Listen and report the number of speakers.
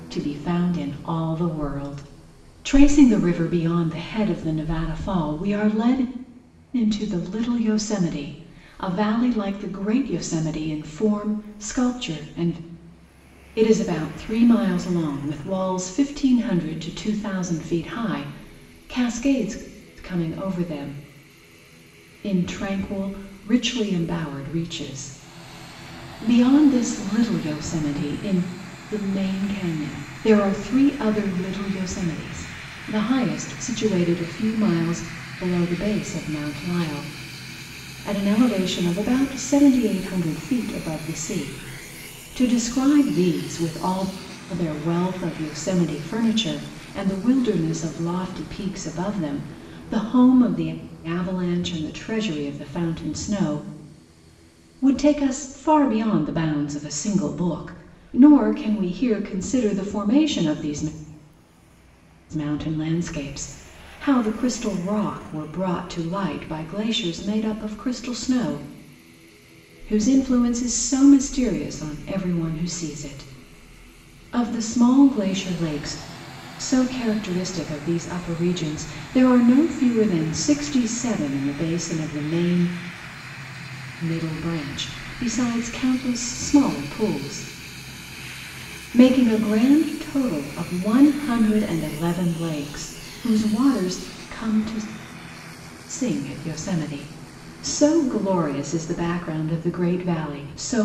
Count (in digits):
1